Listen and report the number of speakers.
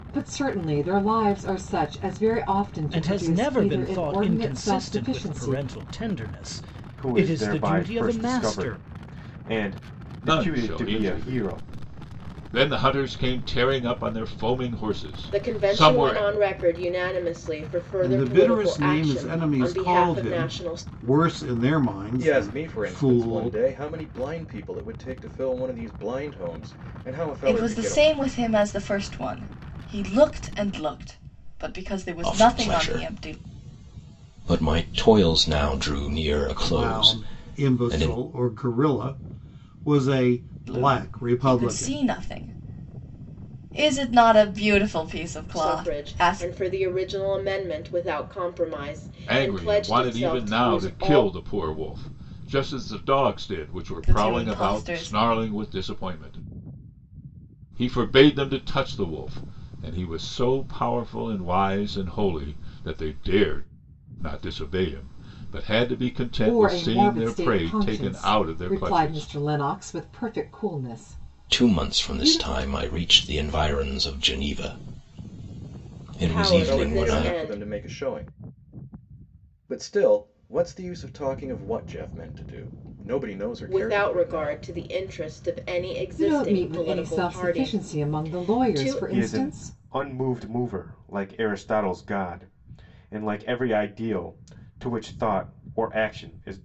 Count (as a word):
nine